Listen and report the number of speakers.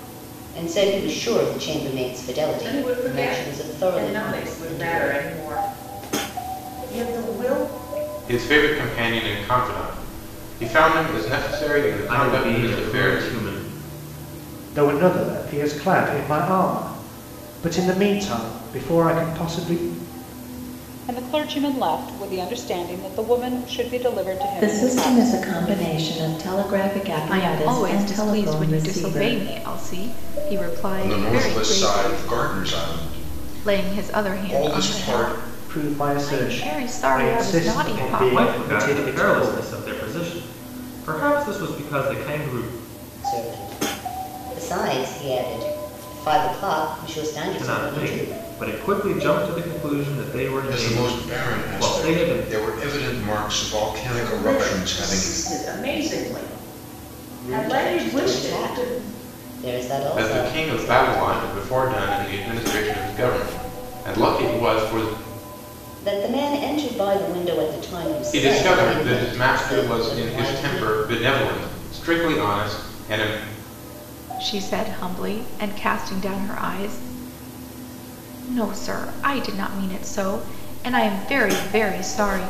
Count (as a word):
ten